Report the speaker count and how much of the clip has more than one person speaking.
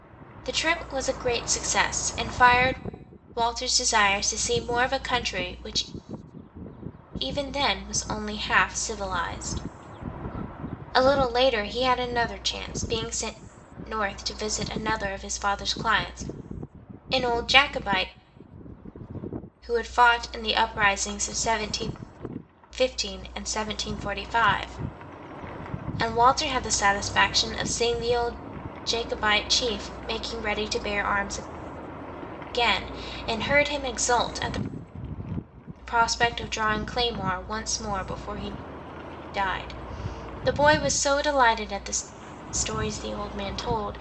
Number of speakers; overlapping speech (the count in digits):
1, no overlap